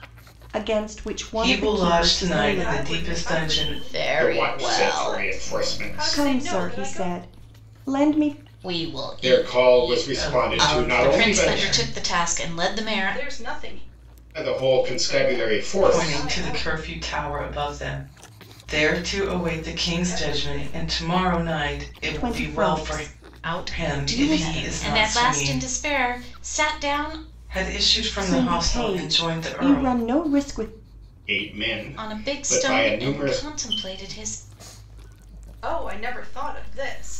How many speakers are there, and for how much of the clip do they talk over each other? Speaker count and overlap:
5, about 51%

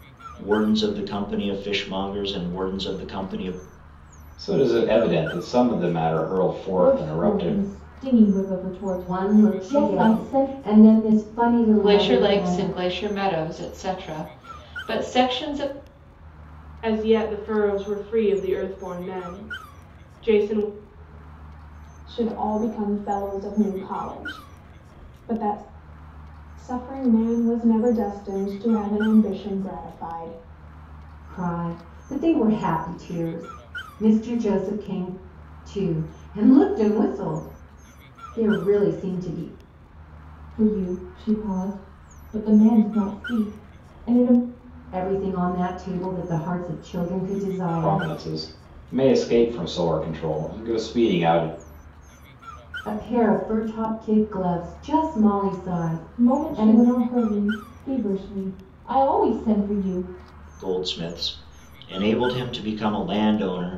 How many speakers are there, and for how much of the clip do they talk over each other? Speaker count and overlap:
7, about 7%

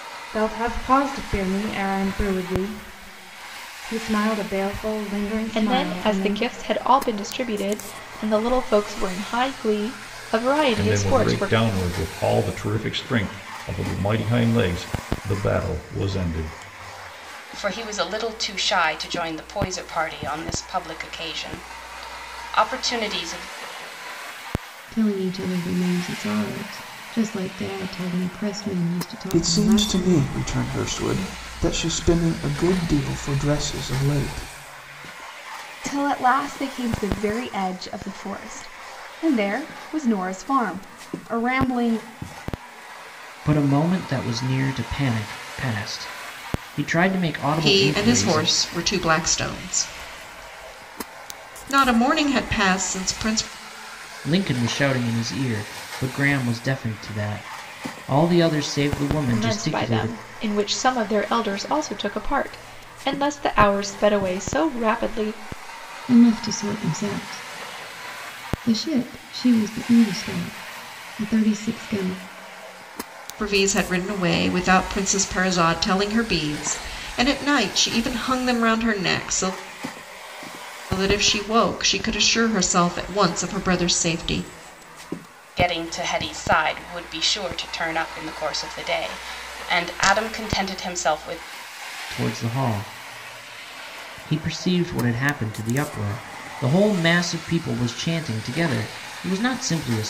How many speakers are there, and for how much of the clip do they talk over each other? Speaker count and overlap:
9, about 5%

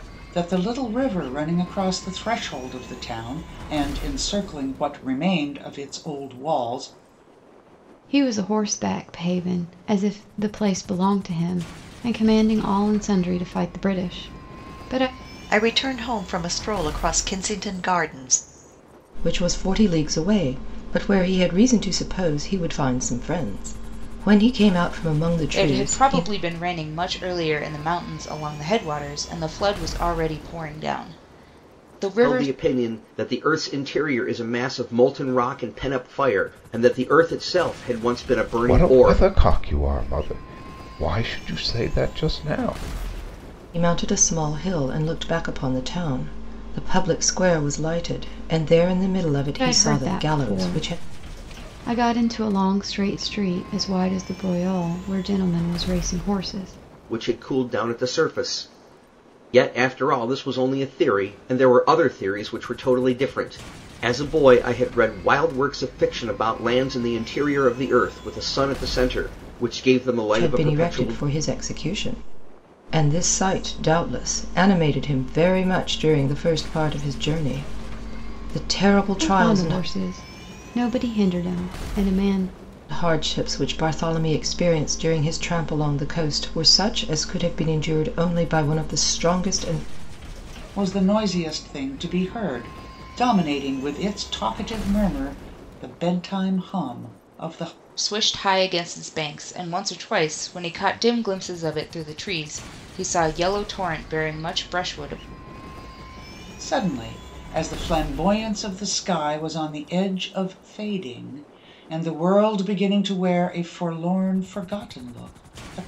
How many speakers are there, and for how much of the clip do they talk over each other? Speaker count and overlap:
7, about 4%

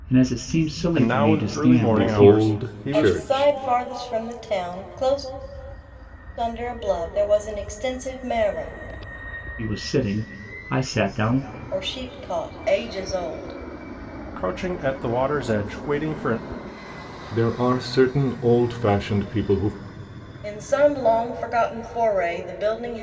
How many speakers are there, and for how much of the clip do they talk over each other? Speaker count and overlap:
4, about 11%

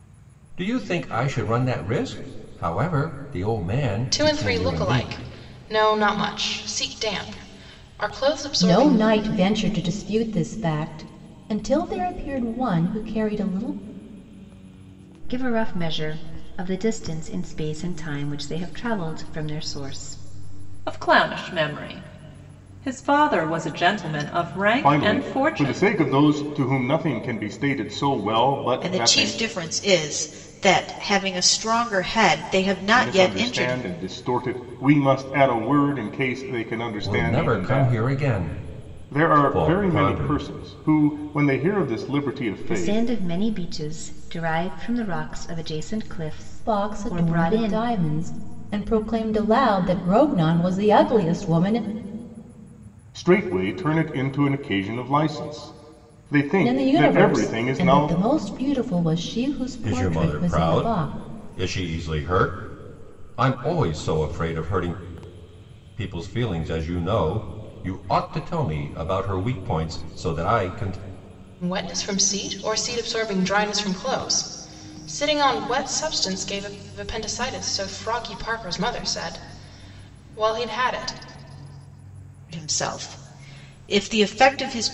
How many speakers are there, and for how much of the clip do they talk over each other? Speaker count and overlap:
7, about 13%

